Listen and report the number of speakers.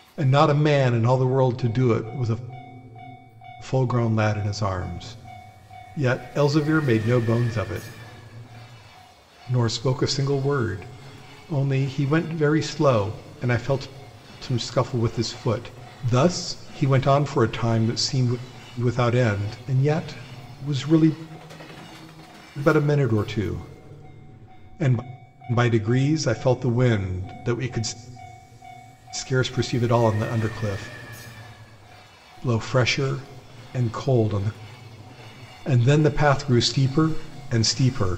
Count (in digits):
1